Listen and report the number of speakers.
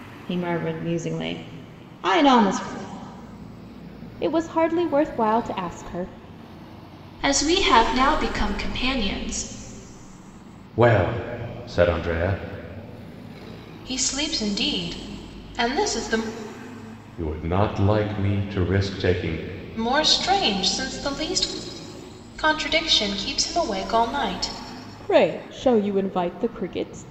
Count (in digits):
5